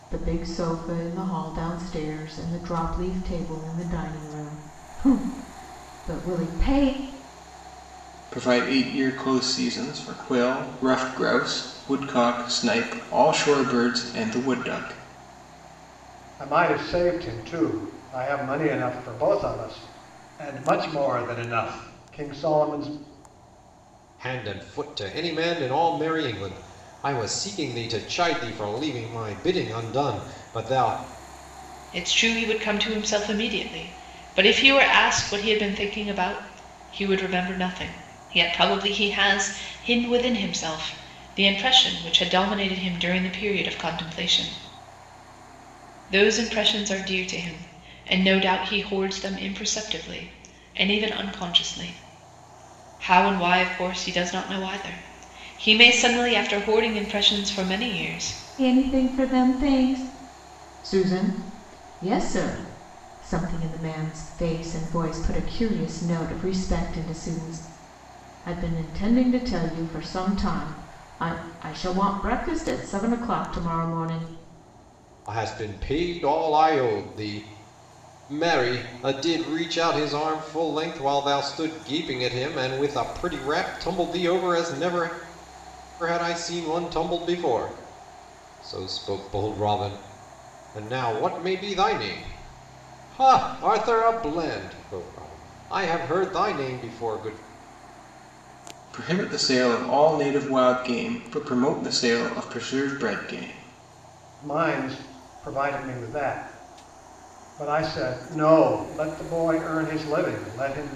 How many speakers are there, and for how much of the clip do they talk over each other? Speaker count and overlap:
5, no overlap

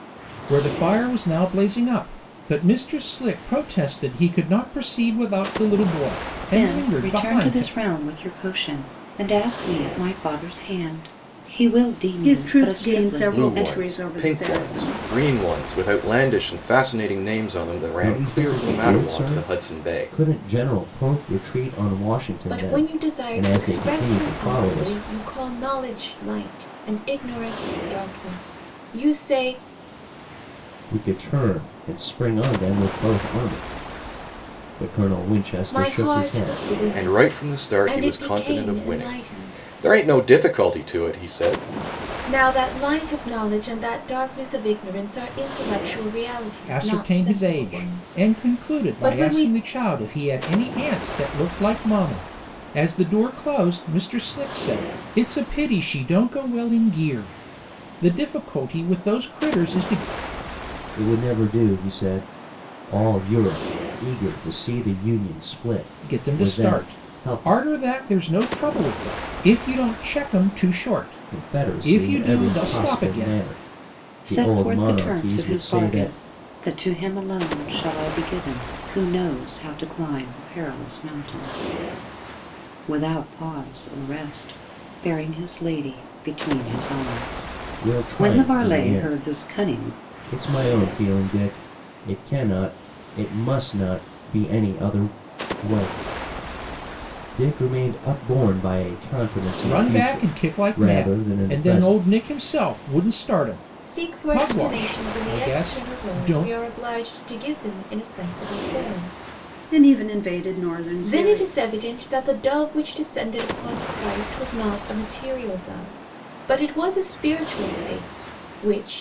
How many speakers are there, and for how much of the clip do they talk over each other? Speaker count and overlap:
6, about 25%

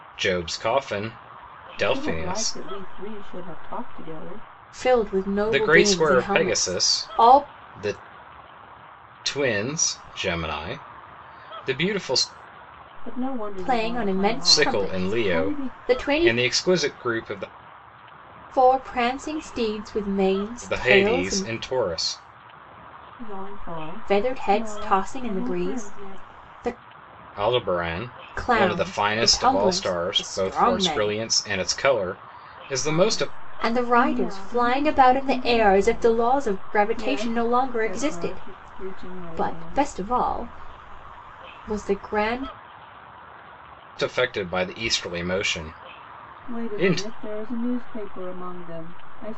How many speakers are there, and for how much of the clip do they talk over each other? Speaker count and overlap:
3, about 38%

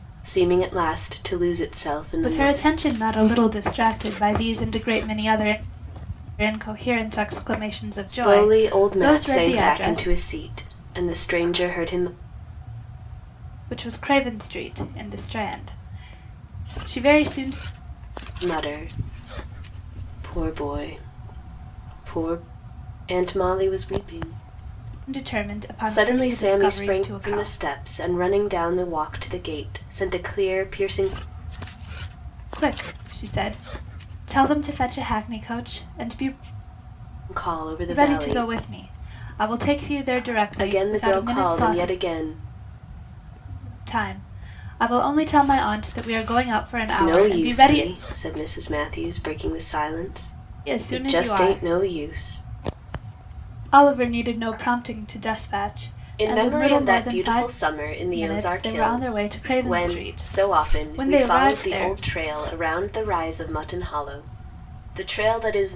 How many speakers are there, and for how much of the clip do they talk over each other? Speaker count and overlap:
2, about 22%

